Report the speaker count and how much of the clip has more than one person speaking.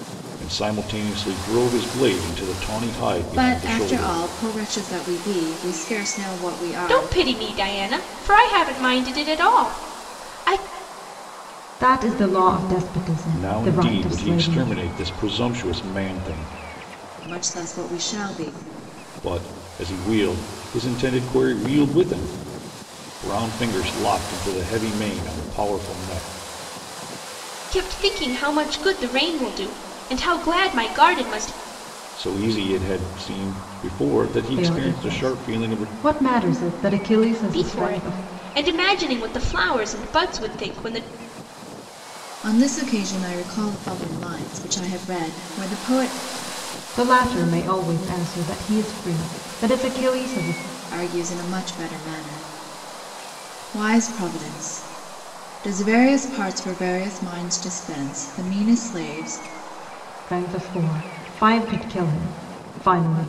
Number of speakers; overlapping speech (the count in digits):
4, about 8%